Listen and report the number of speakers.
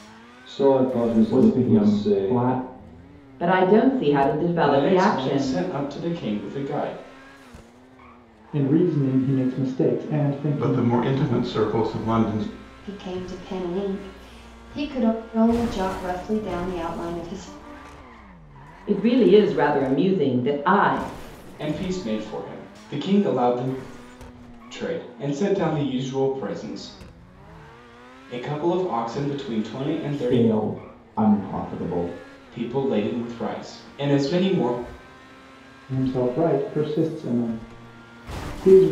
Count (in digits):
7